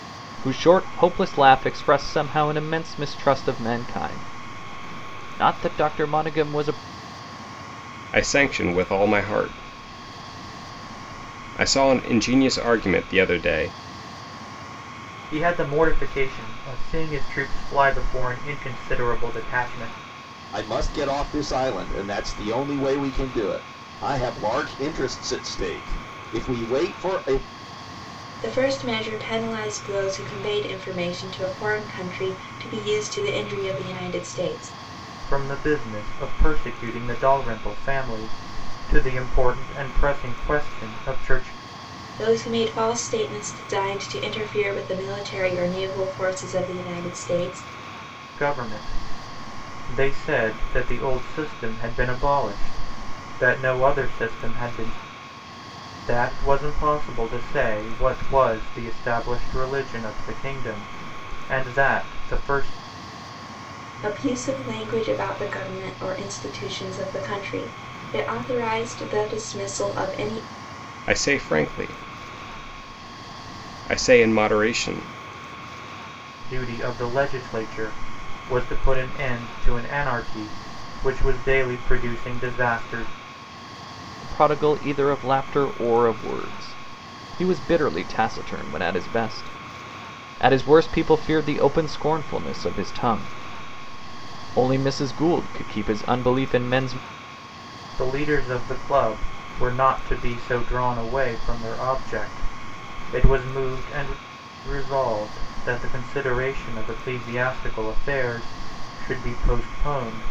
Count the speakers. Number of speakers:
five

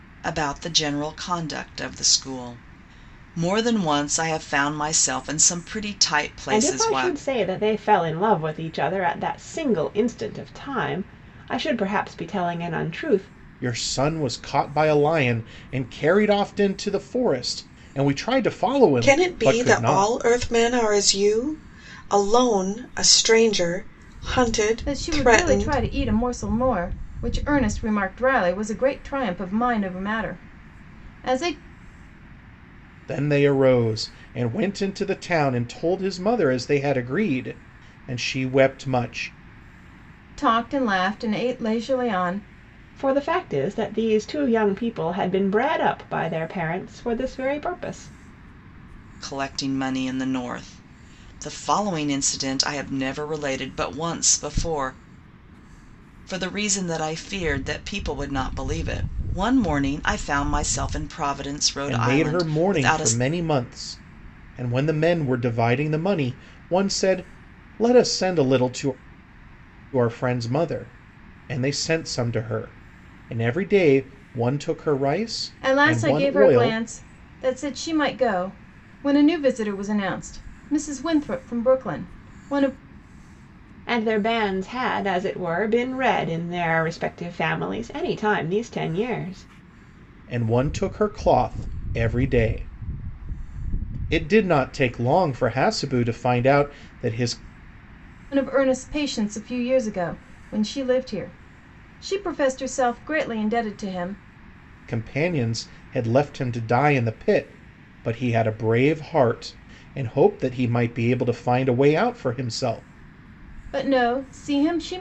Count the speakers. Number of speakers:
five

